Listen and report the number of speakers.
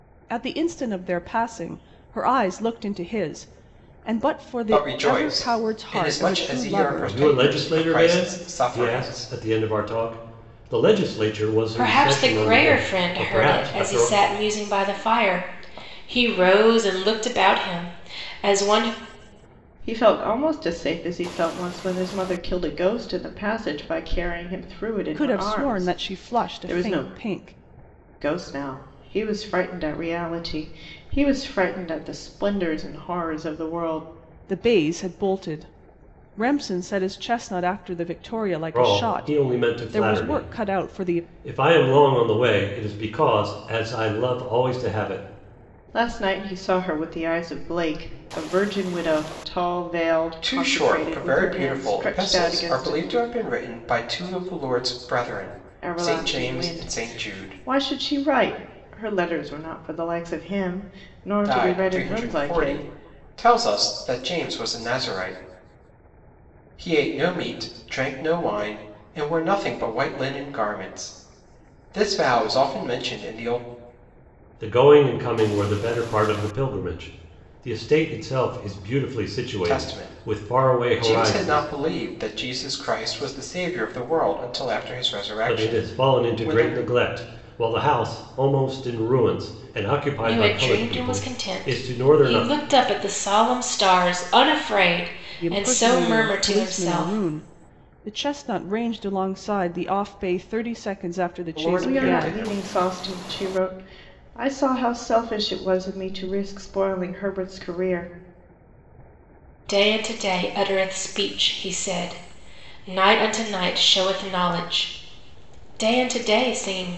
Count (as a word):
five